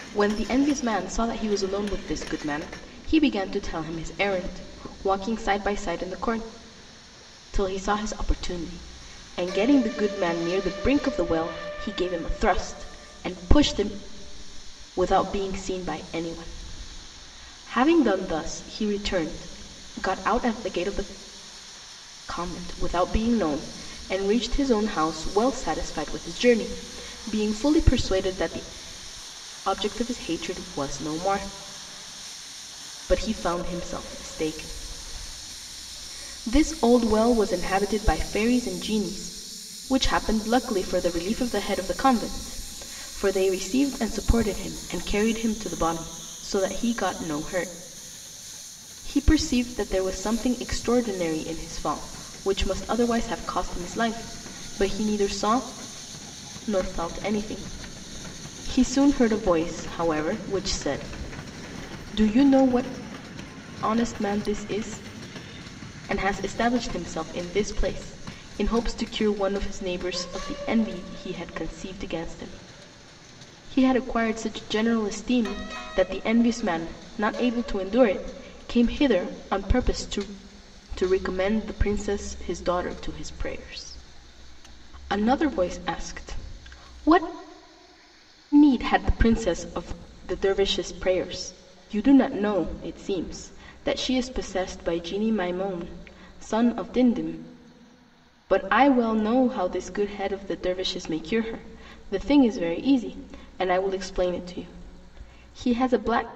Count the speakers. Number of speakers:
1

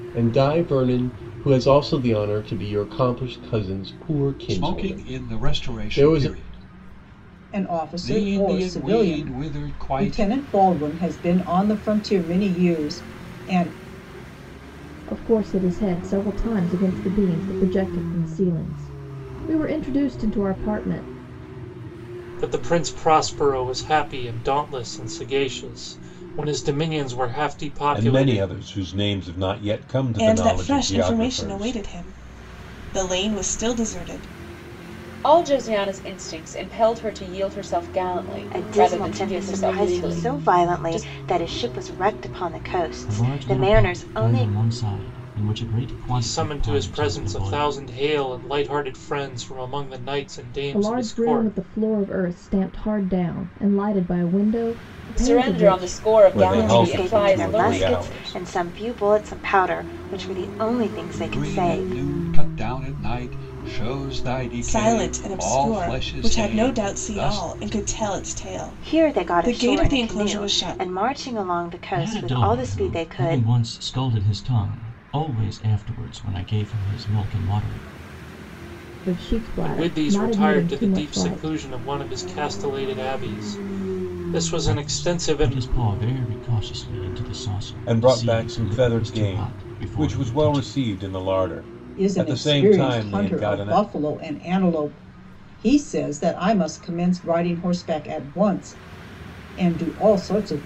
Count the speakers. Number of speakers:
10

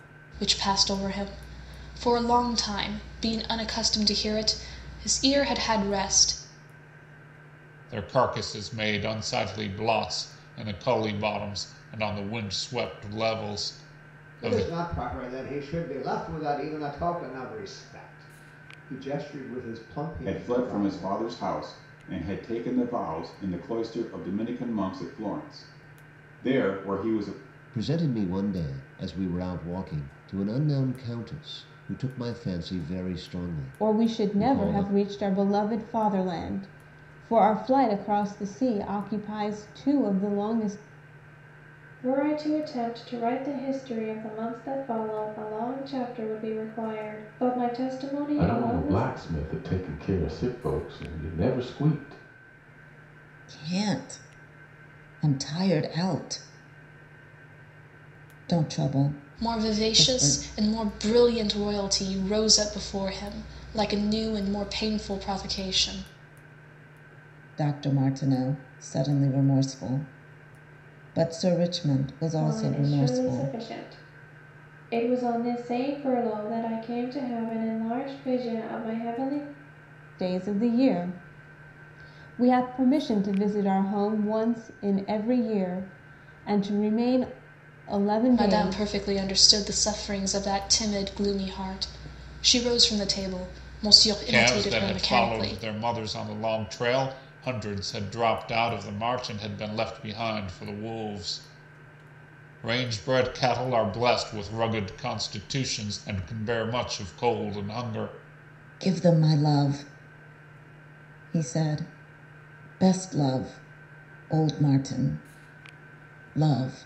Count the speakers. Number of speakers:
9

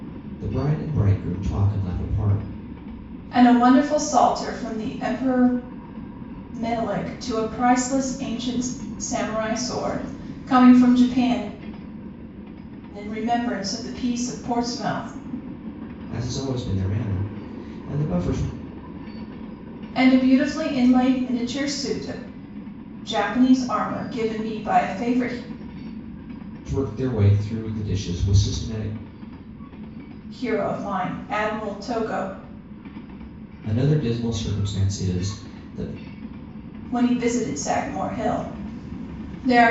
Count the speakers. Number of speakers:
2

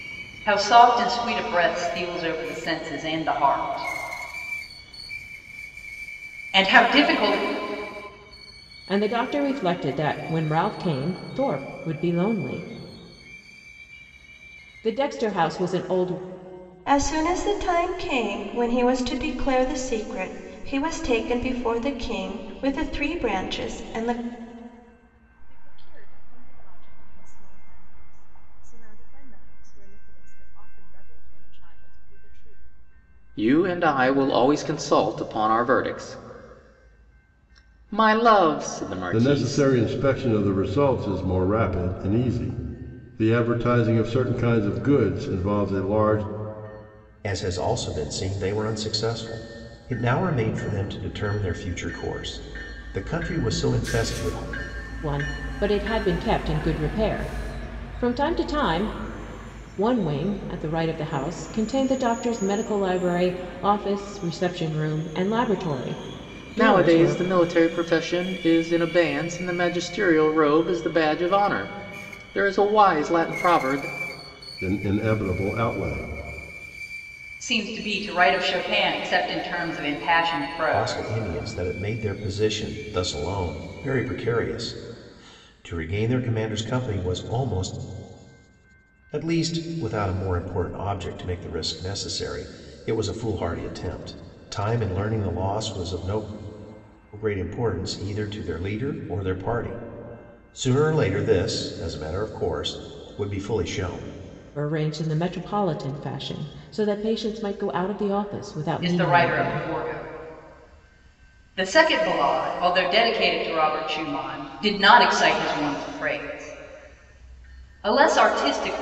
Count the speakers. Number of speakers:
7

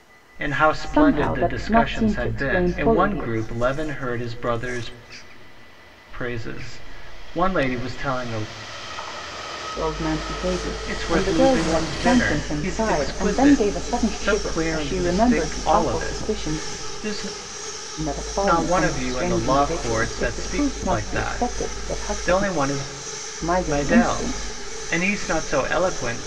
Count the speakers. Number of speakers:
2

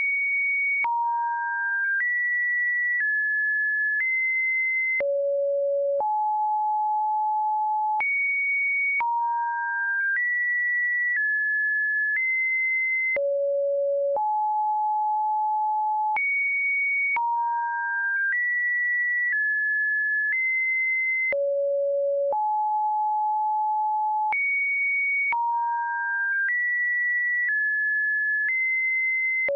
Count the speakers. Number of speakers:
0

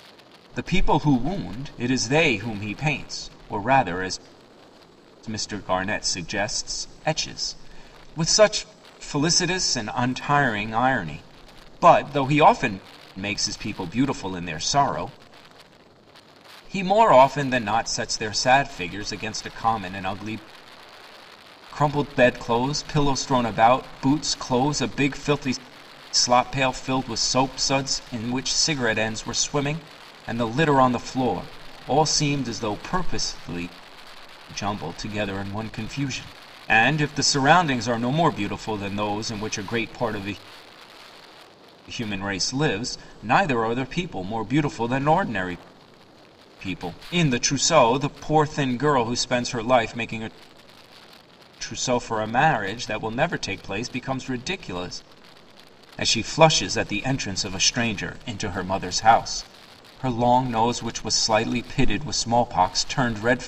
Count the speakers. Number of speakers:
1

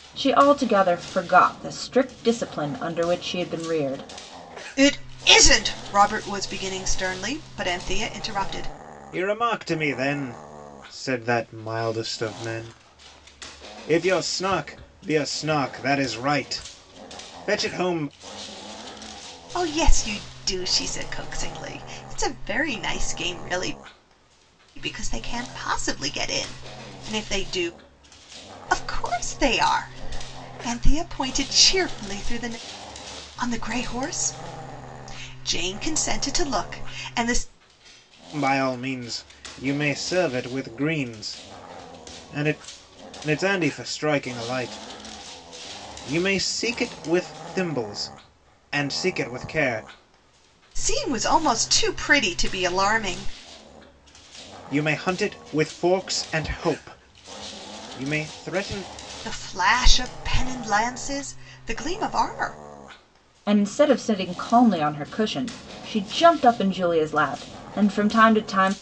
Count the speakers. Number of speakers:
3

